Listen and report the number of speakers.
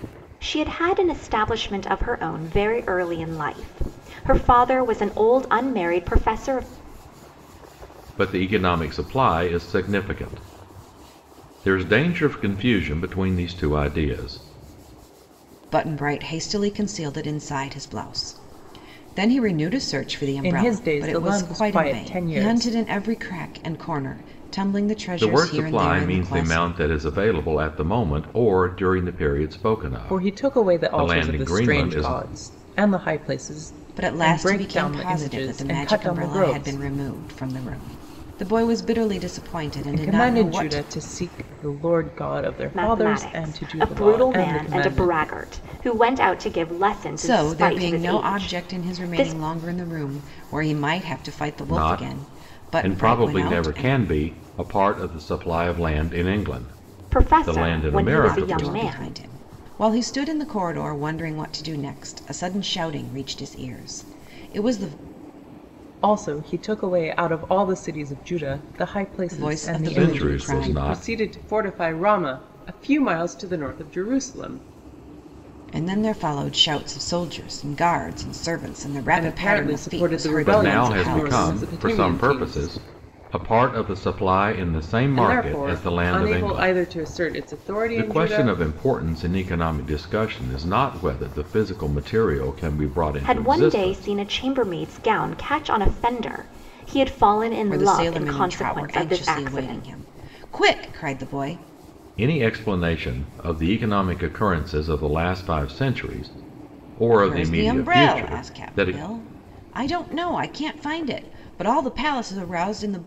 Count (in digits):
4